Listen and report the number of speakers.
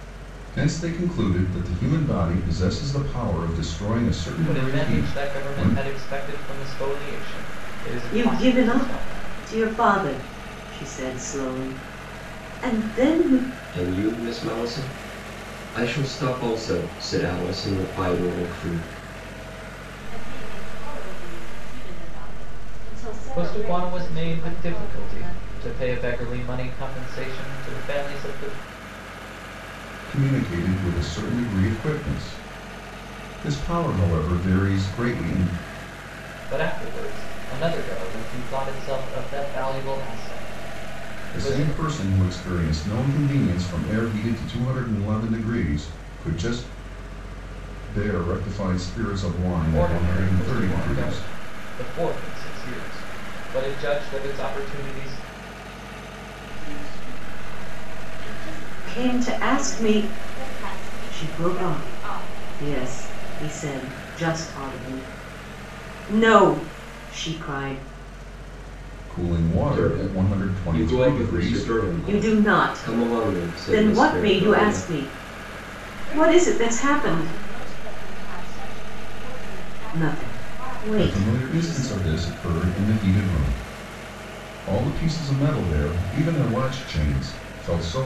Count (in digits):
5